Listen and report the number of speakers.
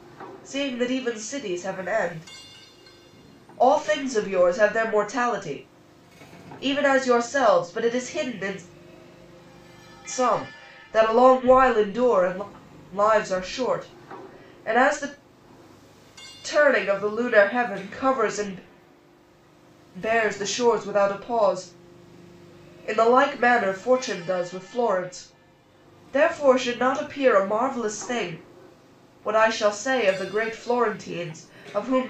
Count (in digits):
1